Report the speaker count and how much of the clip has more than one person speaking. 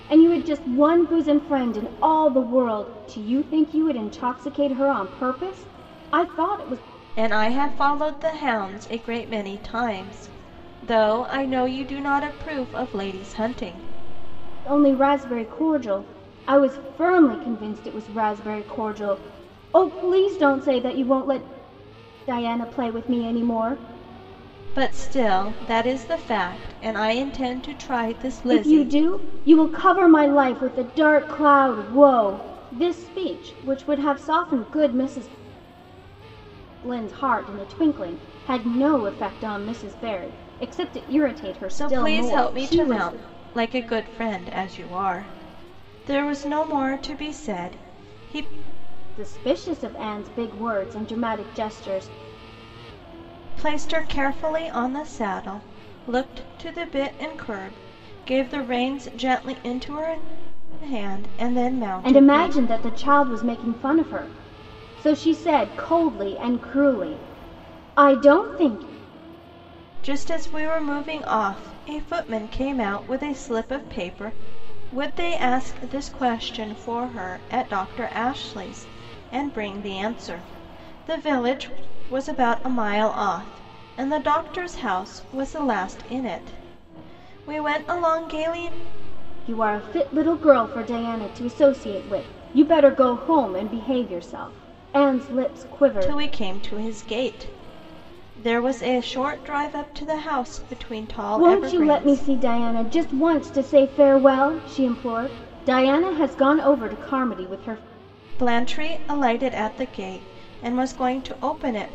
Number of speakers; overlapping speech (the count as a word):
two, about 3%